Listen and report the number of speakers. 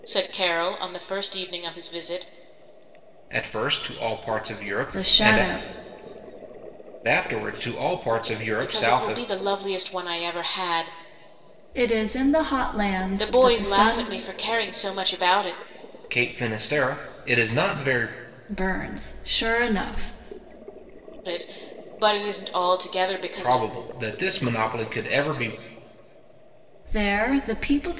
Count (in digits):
3